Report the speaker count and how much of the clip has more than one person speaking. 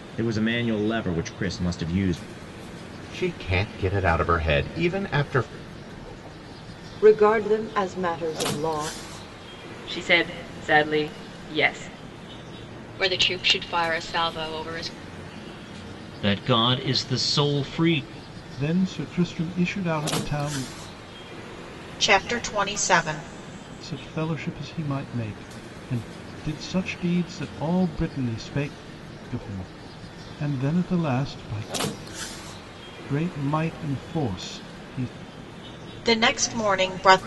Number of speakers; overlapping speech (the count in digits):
8, no overlap